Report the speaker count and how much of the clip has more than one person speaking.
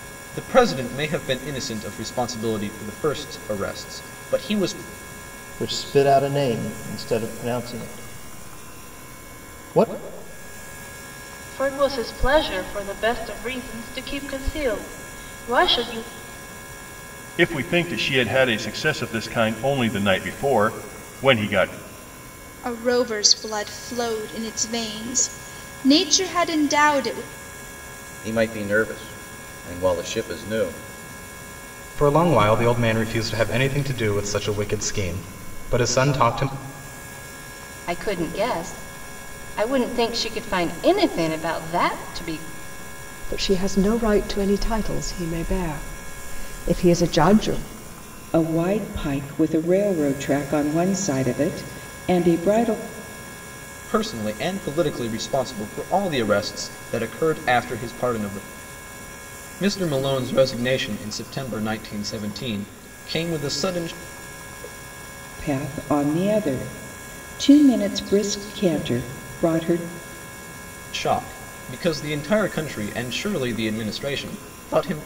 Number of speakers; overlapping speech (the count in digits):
10, no overlap